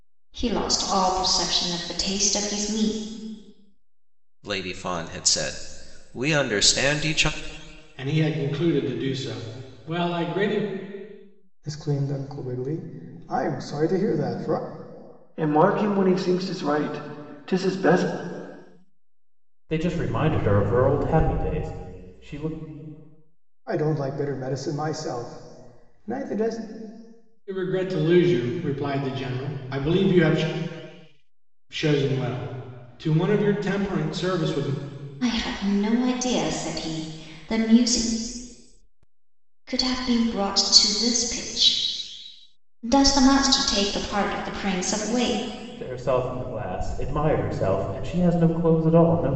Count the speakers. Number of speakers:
six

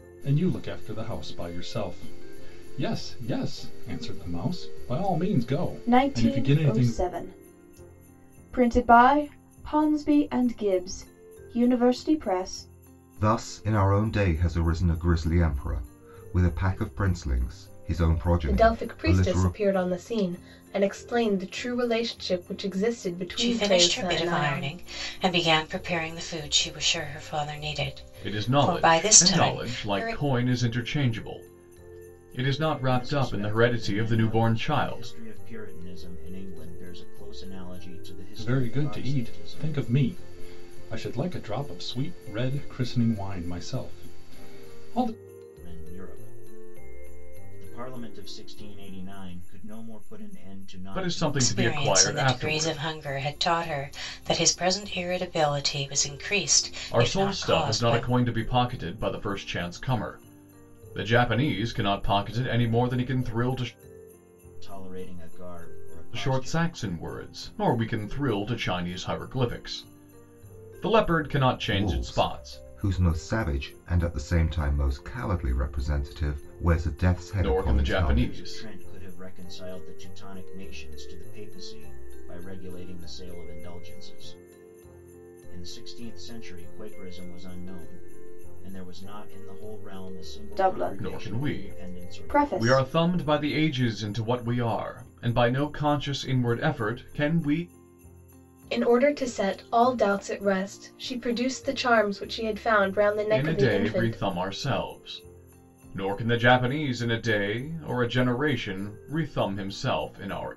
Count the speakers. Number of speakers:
seven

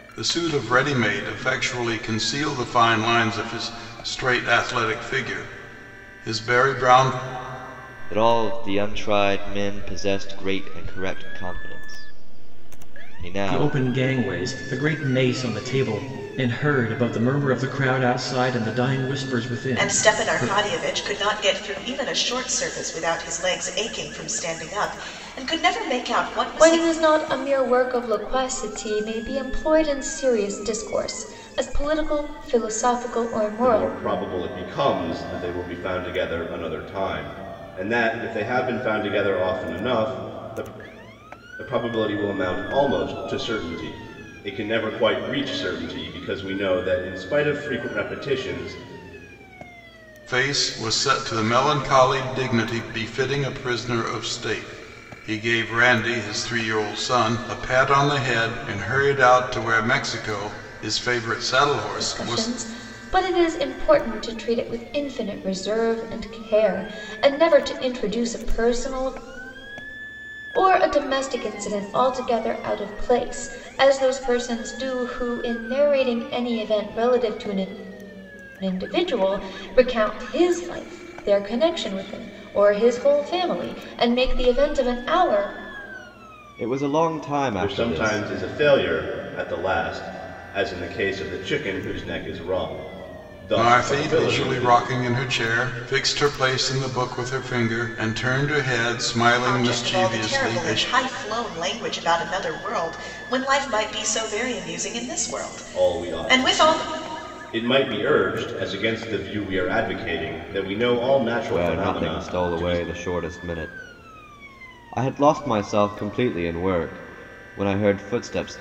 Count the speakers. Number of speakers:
six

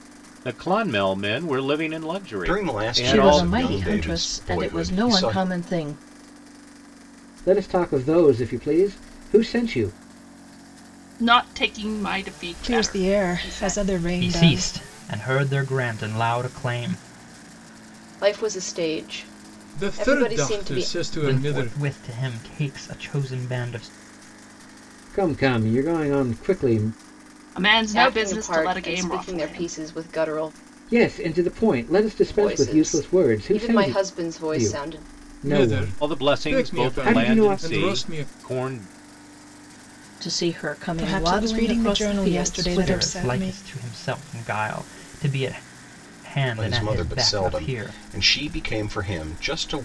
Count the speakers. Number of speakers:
nine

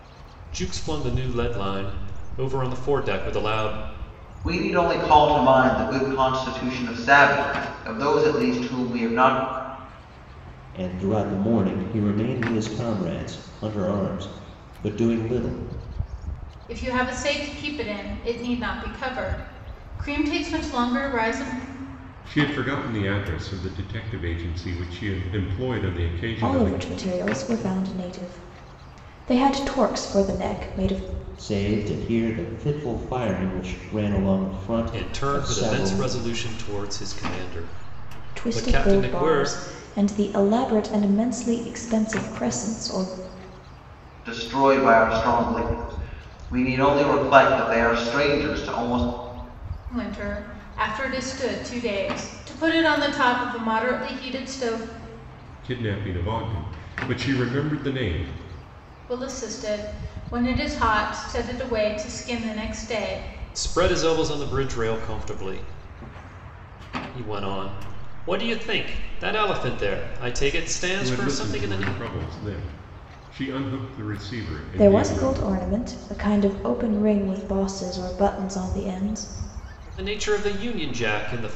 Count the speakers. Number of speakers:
six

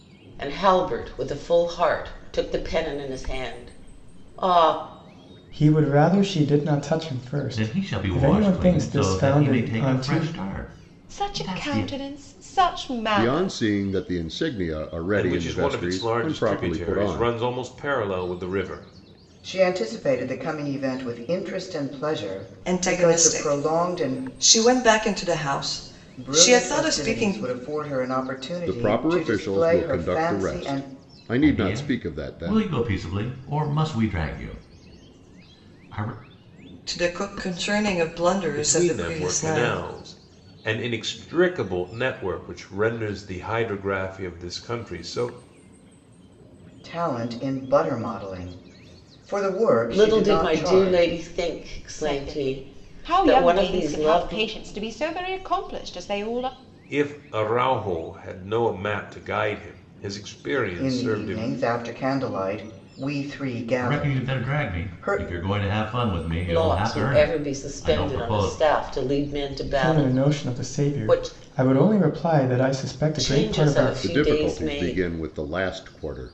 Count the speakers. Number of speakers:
eight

